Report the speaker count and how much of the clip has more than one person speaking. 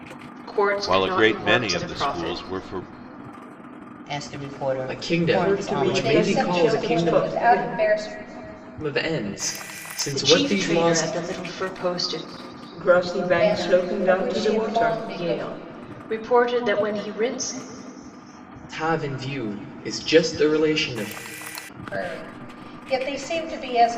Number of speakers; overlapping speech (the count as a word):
six, about 33%